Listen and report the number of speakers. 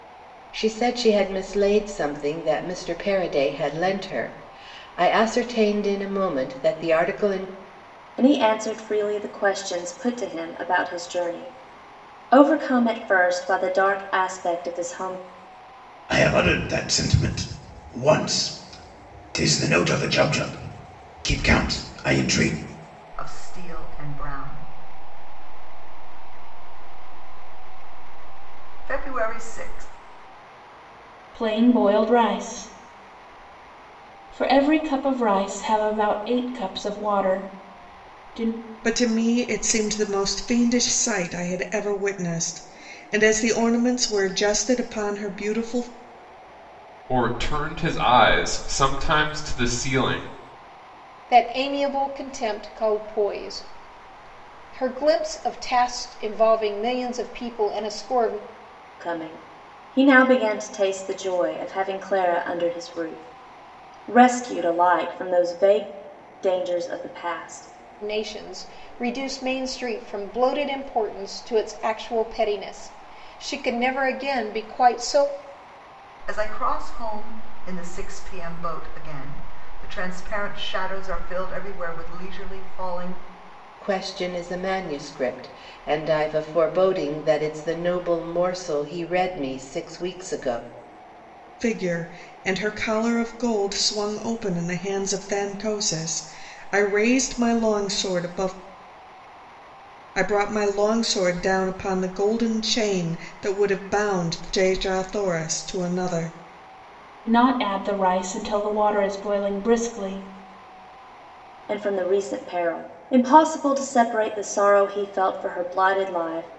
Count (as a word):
eight